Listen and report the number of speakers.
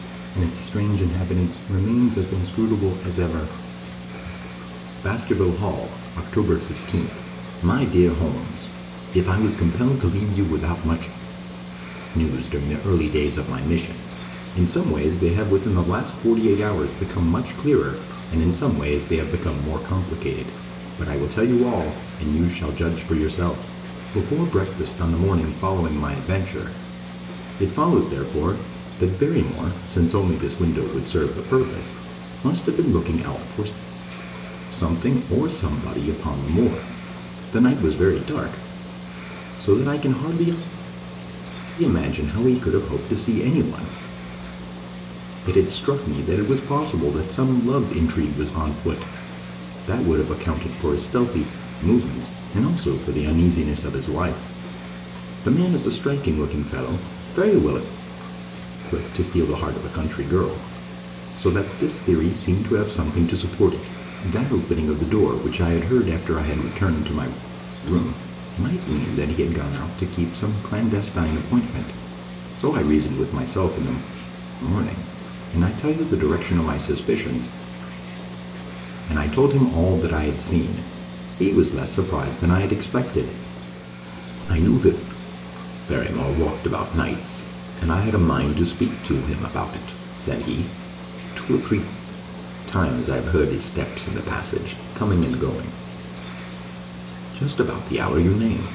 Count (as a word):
one